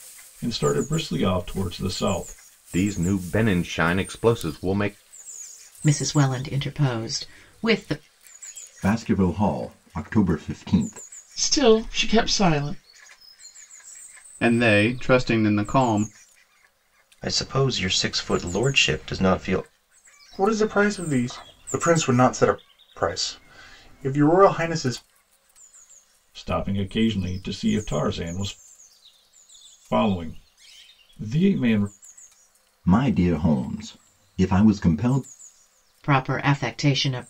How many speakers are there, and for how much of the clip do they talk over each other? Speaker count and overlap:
eight, no overlap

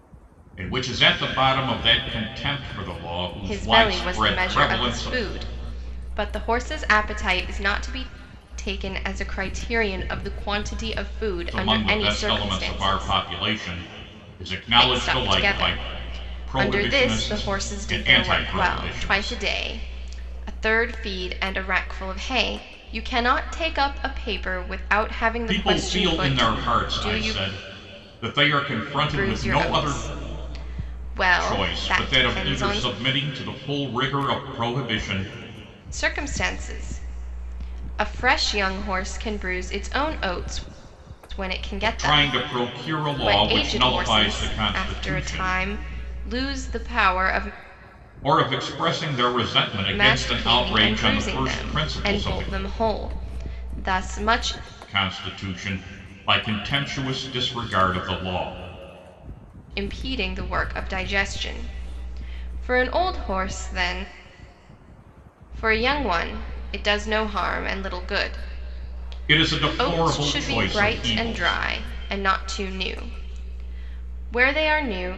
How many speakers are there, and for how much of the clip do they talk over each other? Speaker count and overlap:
two, about 27%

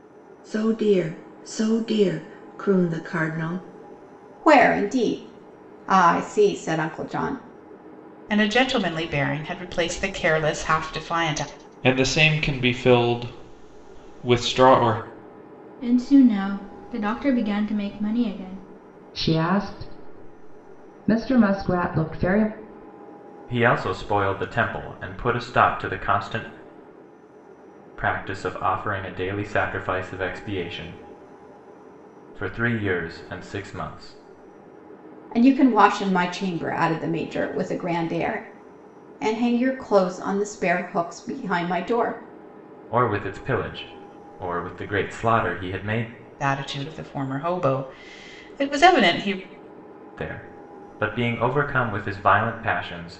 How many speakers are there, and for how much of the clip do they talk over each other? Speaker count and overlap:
seven, no overlap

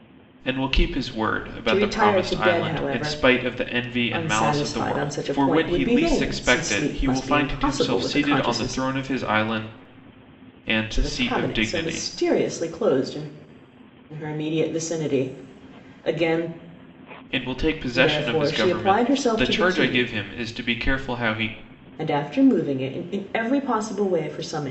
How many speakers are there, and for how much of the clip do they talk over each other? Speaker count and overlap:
two, about 38%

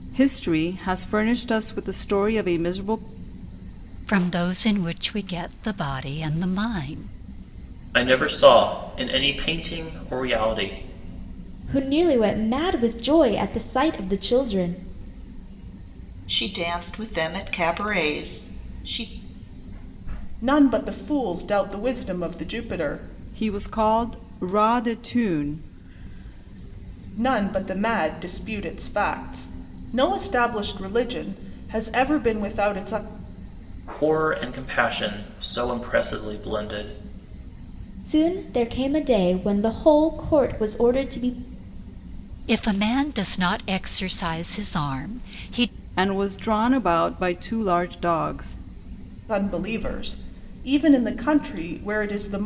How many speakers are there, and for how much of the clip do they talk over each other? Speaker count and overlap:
six, no overlap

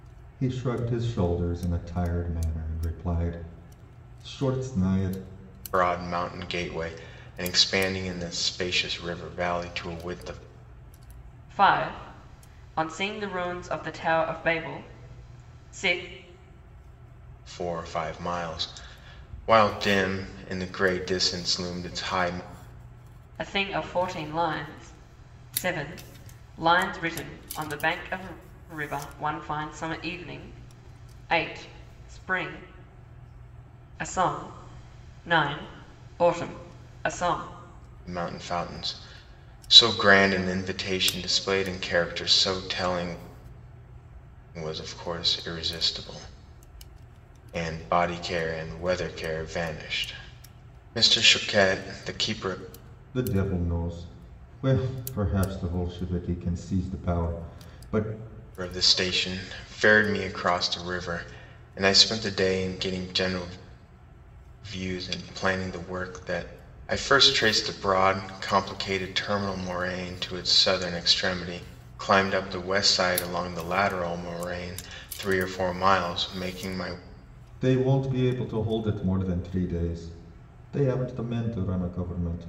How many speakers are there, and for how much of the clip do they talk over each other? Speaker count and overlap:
three, no overlap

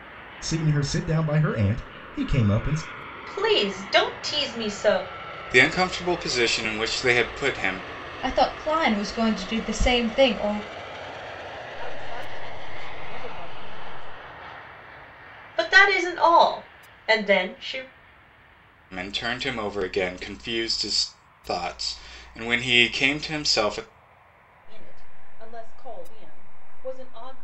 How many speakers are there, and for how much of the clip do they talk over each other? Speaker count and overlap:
five, no overlap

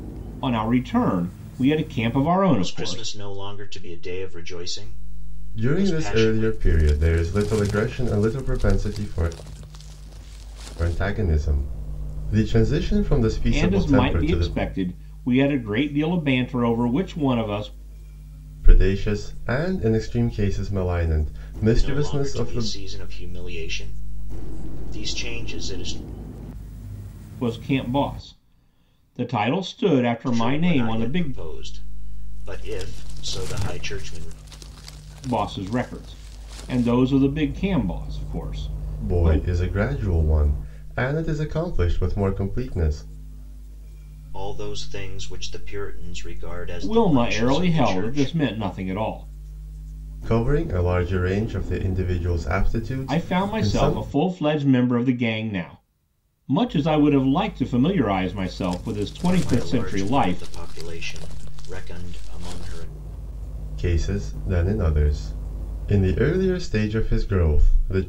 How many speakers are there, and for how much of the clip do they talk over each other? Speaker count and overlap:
three, about 13%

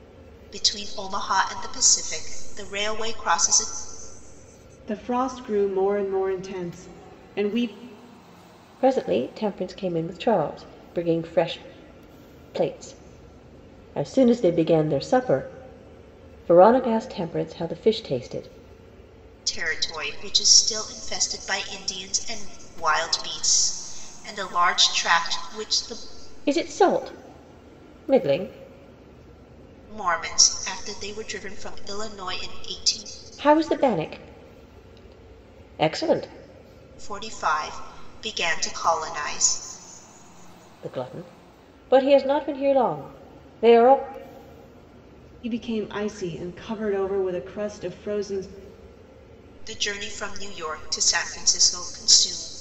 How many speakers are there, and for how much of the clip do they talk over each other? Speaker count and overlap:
three, no overlap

